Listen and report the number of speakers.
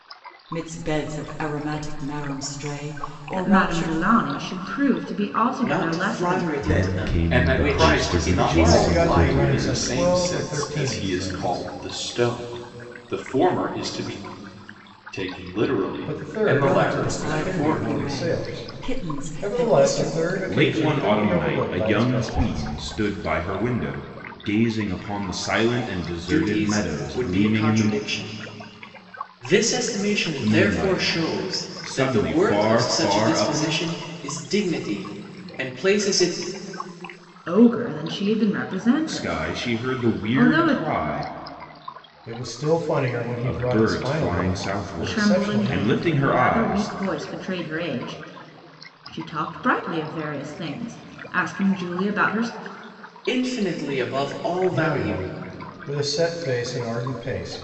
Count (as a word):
six